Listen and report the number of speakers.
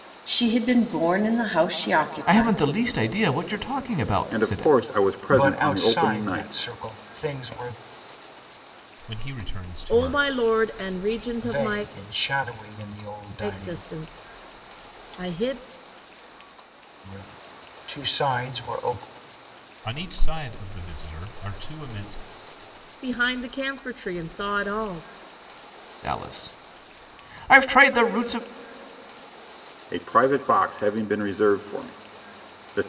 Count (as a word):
six